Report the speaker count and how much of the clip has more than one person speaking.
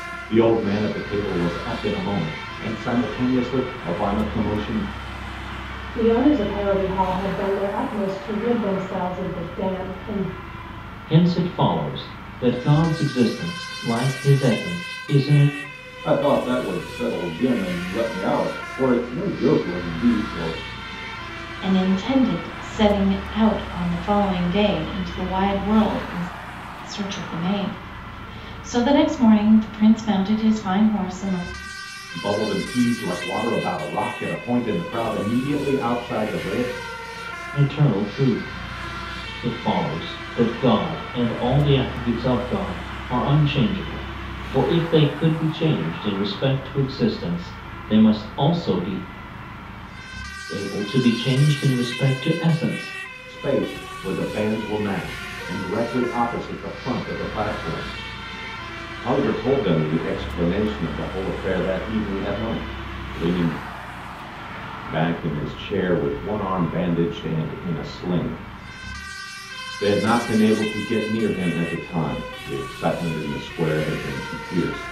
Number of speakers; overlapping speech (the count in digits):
5, no overlap